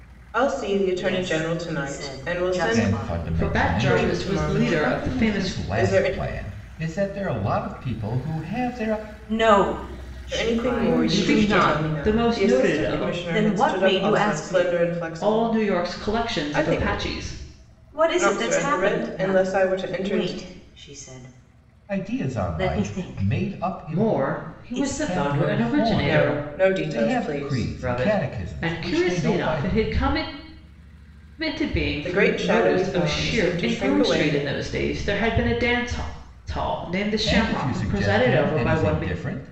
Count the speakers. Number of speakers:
four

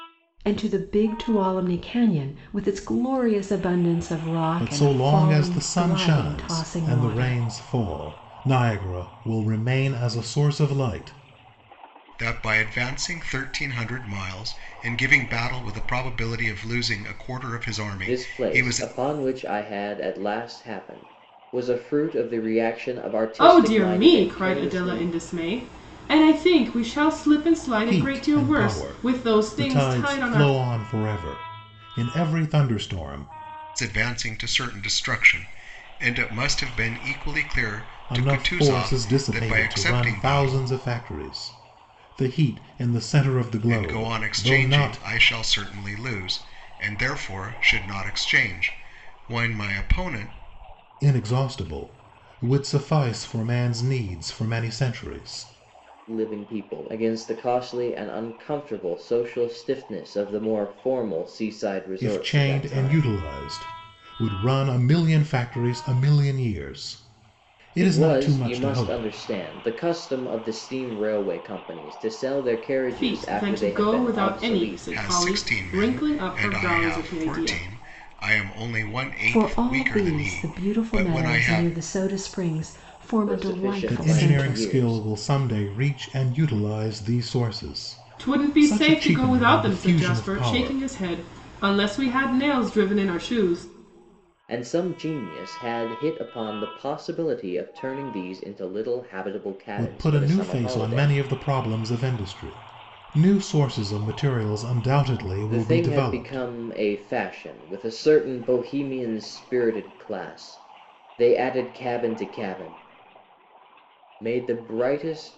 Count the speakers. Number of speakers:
five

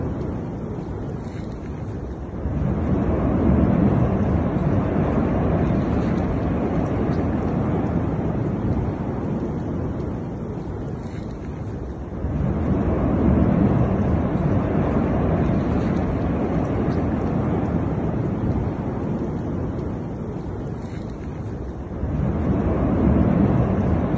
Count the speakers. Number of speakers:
zero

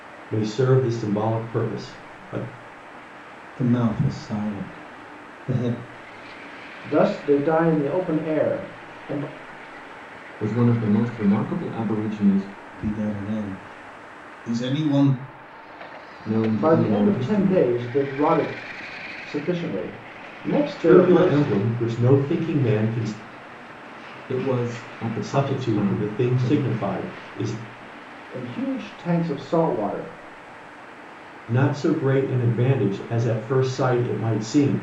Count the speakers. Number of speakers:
four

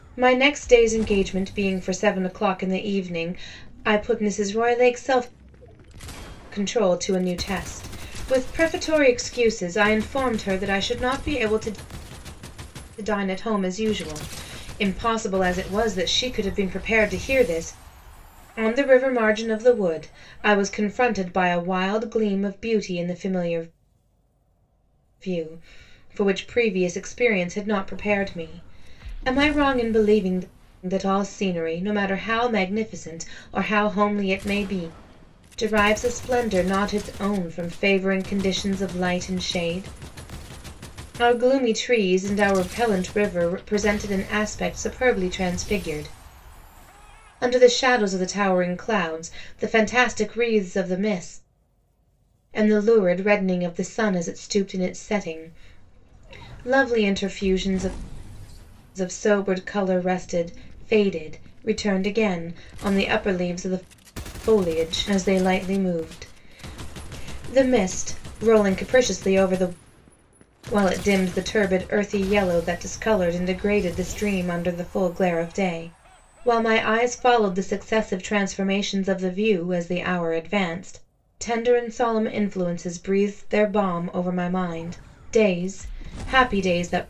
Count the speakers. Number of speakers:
one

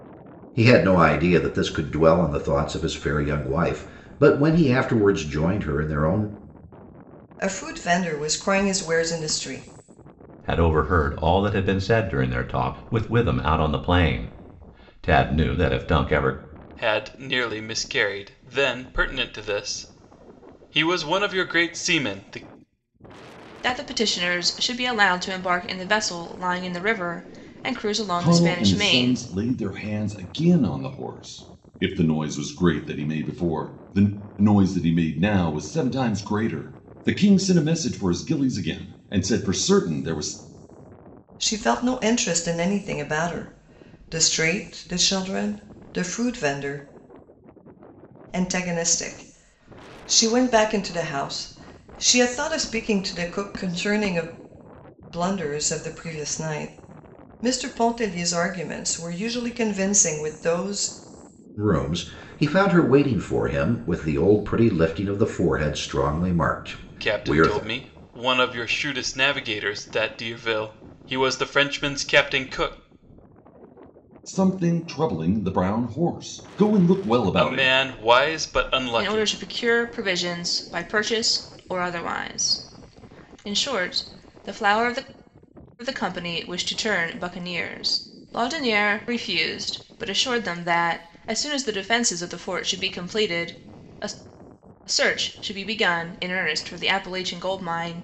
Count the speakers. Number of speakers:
six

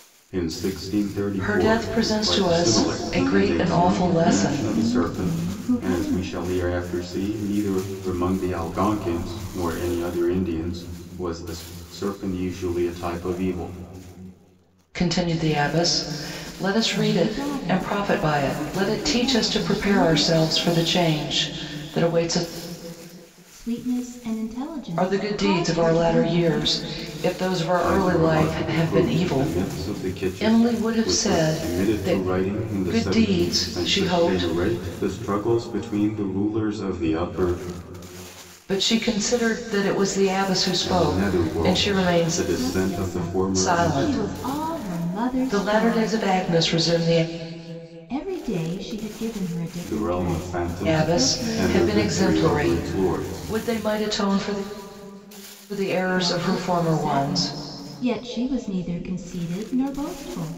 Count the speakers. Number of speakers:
three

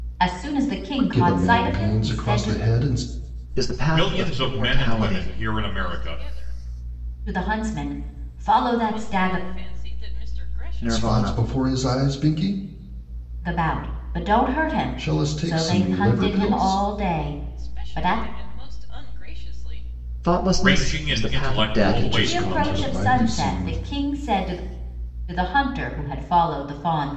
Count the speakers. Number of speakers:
five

